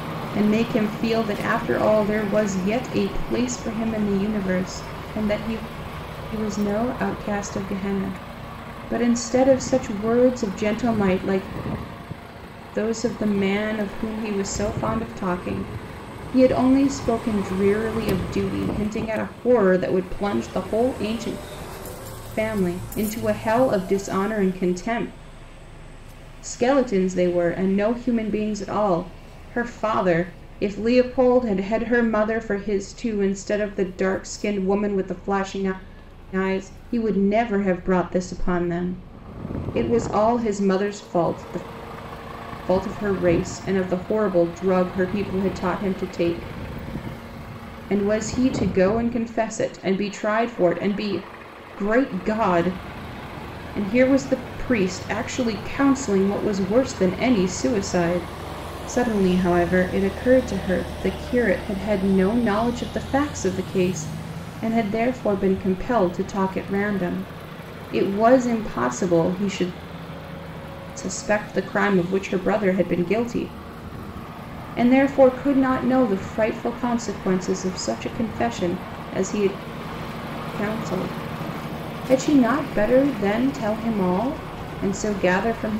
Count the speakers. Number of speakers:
1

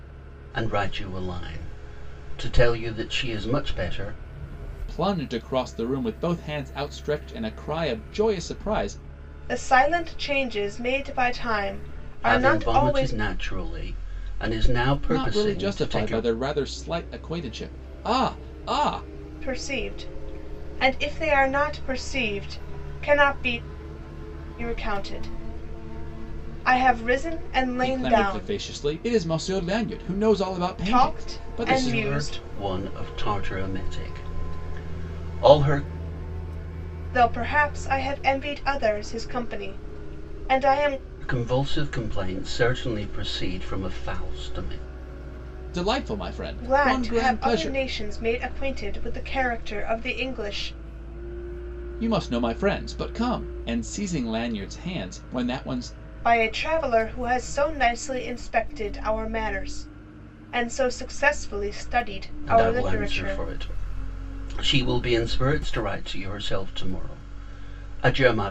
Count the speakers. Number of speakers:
3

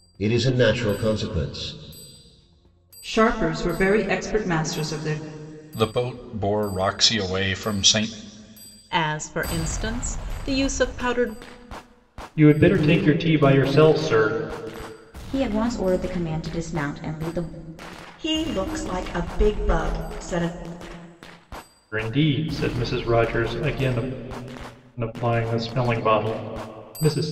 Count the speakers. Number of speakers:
7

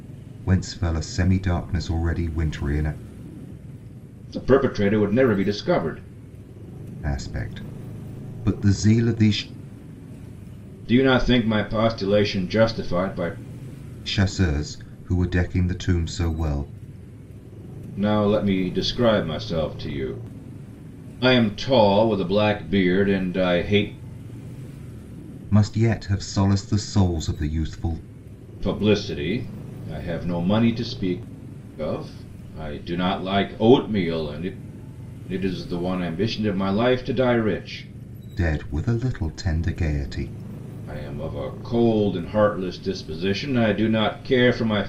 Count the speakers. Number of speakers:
2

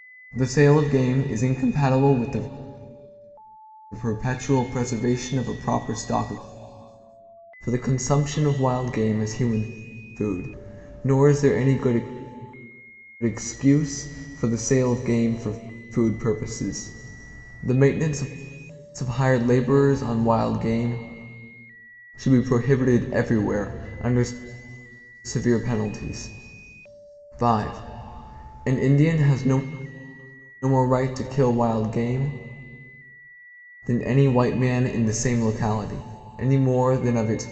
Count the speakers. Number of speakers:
1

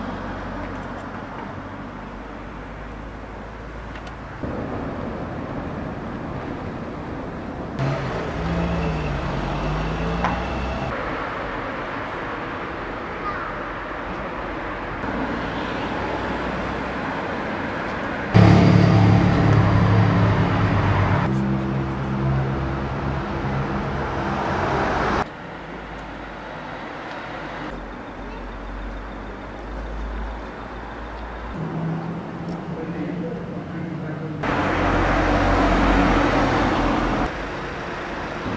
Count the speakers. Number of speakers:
0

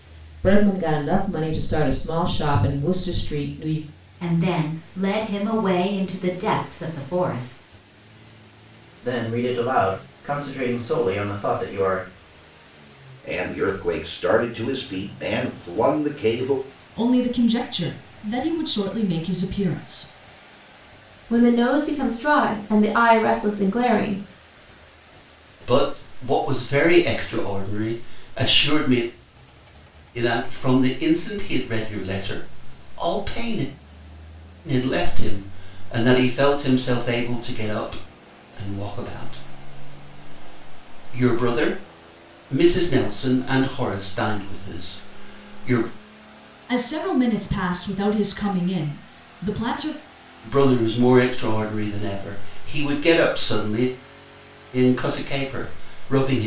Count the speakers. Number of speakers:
7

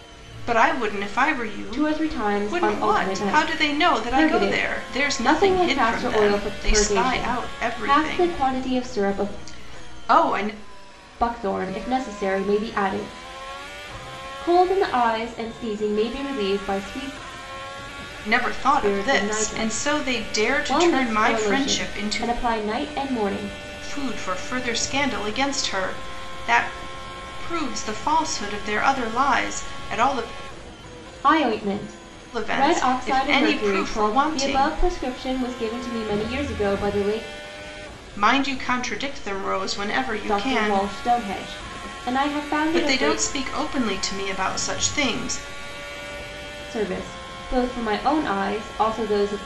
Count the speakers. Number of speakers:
2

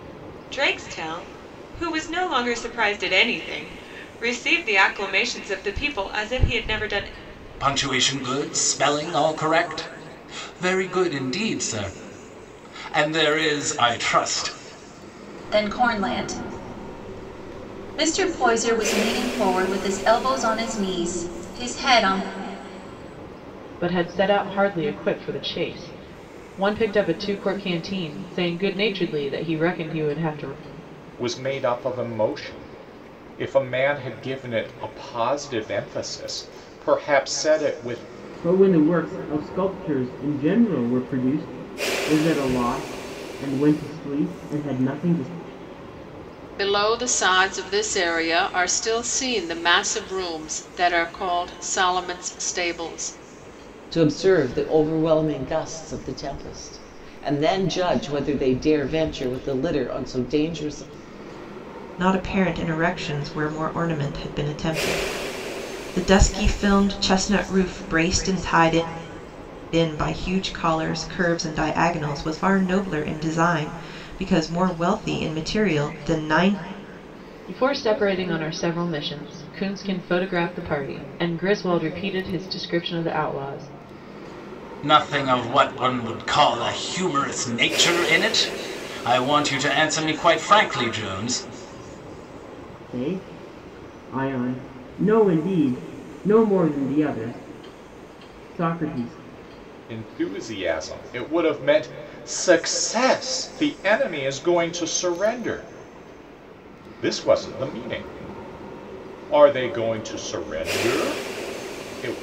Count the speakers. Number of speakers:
9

